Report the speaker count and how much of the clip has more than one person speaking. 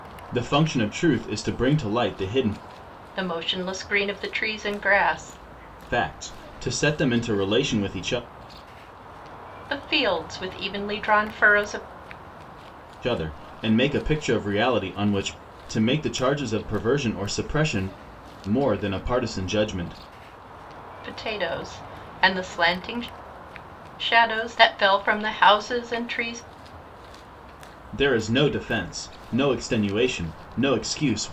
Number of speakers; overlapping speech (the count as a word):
two, no overlap